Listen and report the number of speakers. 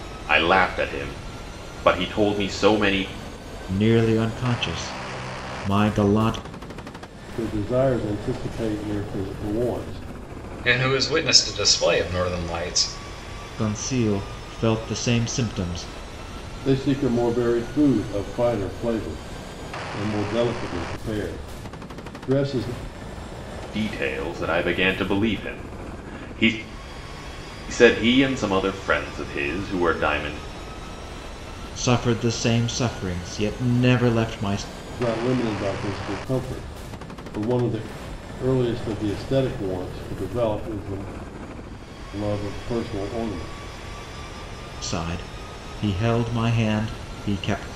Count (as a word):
four